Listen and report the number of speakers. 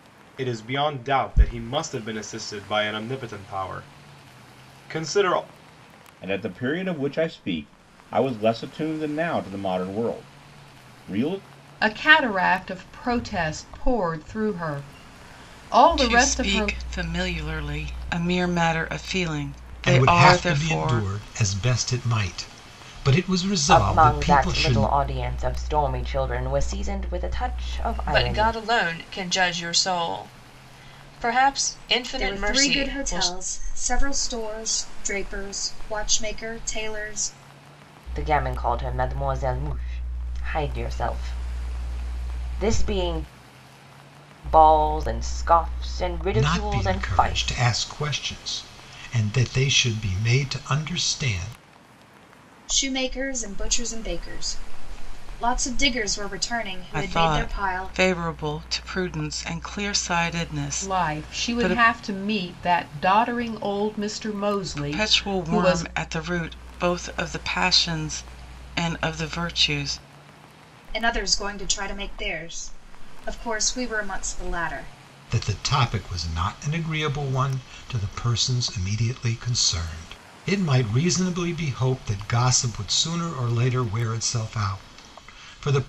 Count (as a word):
eight